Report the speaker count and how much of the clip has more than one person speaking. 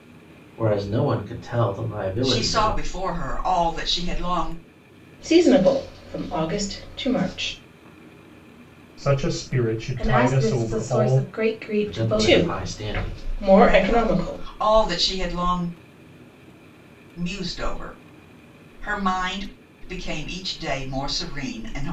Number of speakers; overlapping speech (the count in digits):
5, about 18%